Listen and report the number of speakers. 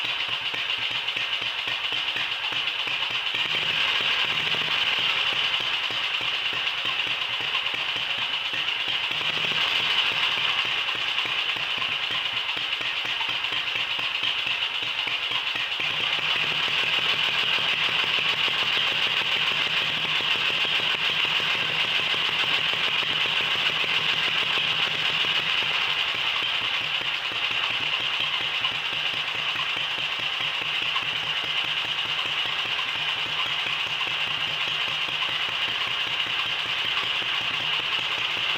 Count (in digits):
0